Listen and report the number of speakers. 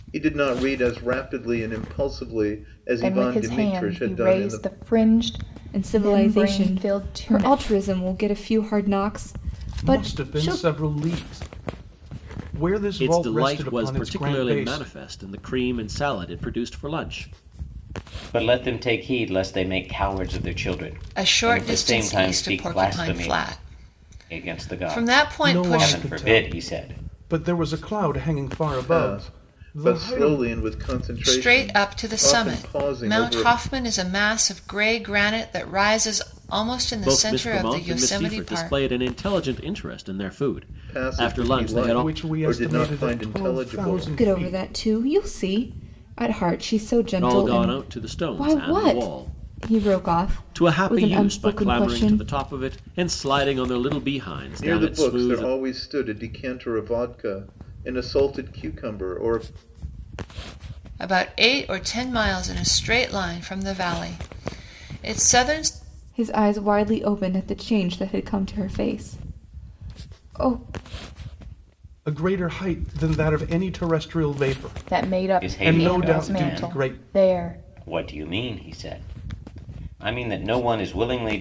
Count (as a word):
seven